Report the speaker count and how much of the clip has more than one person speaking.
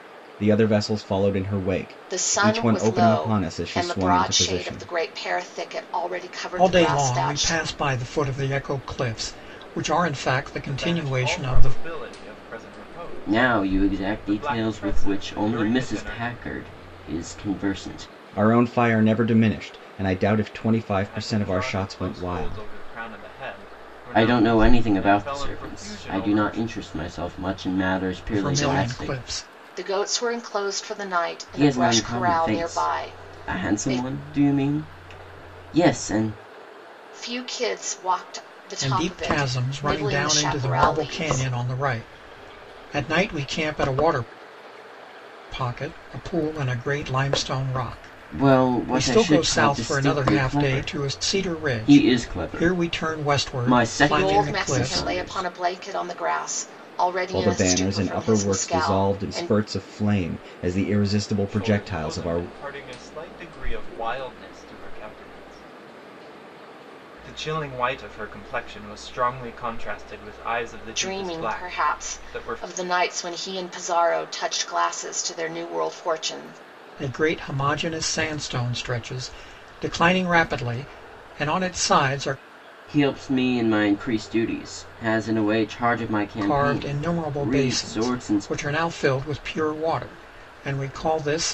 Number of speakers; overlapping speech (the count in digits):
5, about 35%